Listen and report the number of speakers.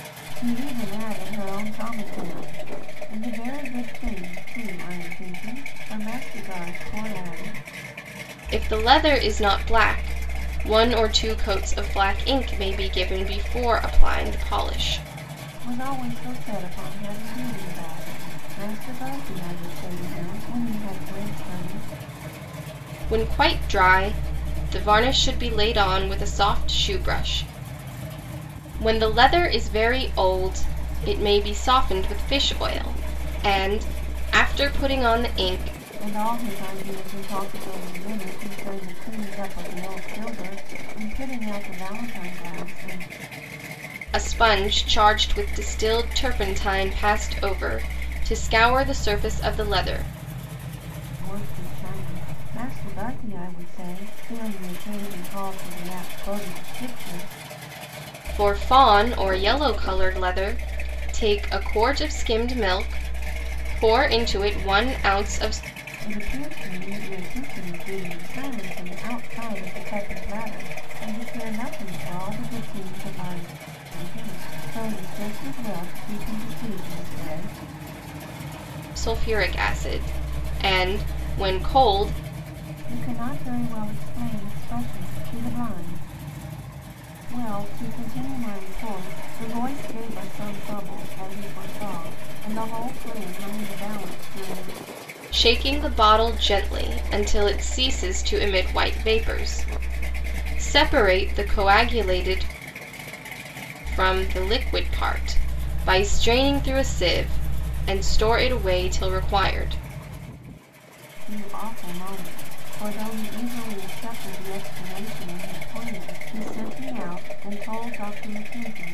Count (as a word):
two